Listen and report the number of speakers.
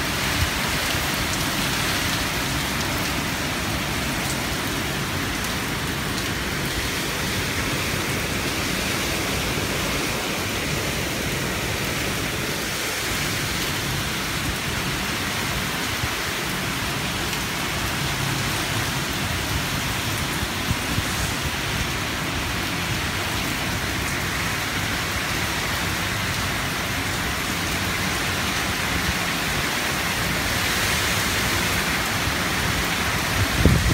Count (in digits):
0